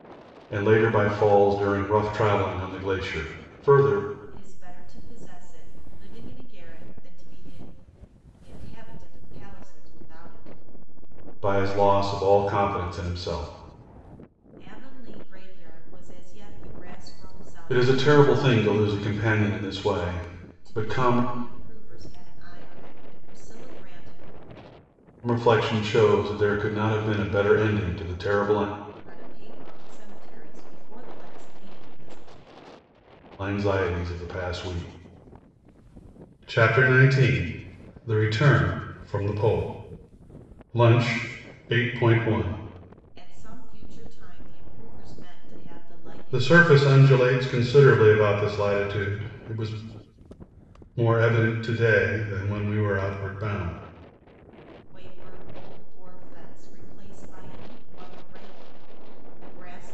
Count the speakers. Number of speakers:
two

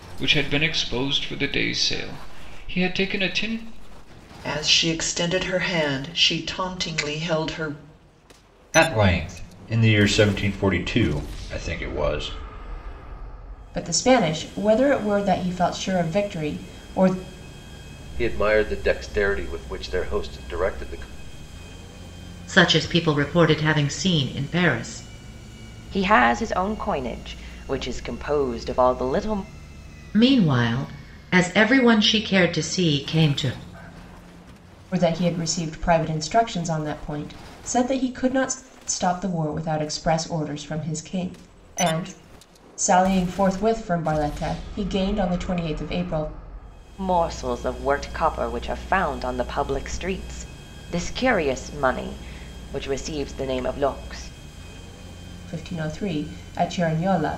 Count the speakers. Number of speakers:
seven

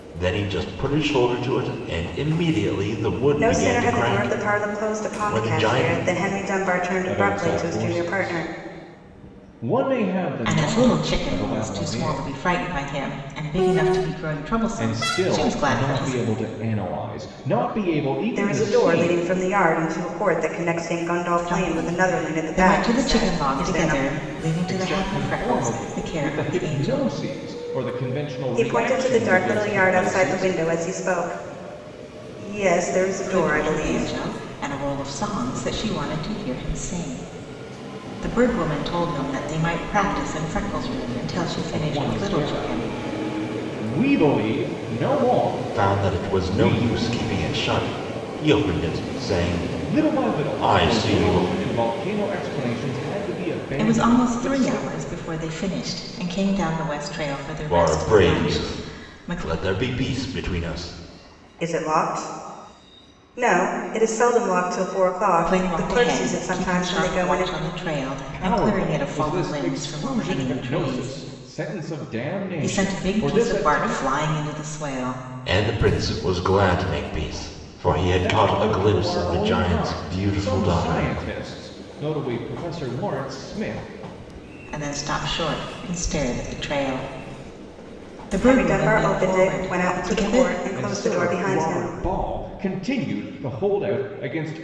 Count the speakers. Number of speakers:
four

